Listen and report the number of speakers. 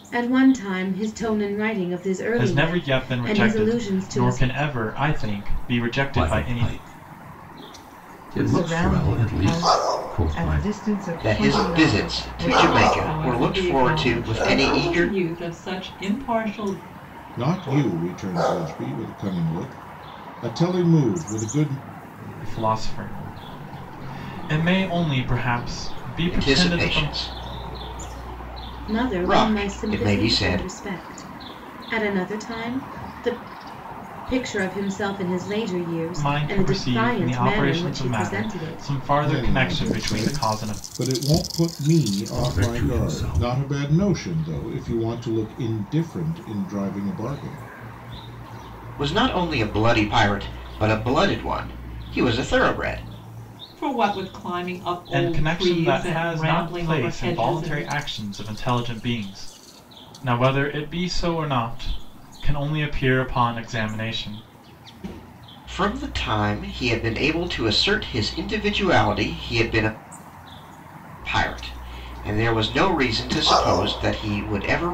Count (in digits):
7